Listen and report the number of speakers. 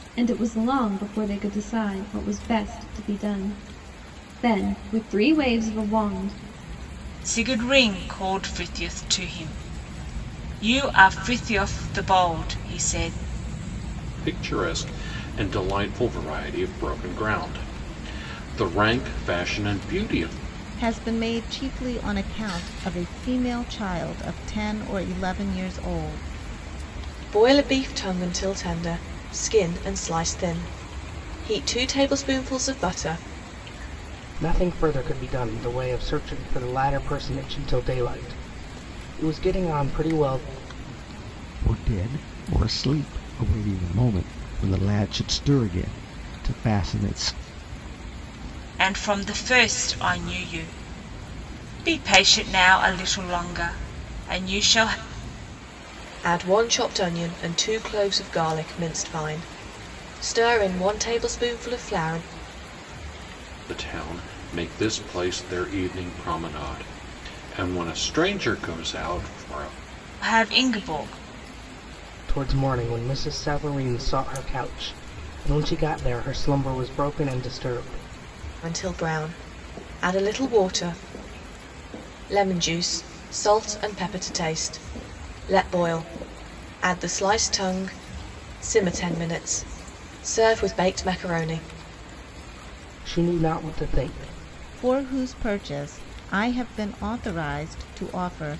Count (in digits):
7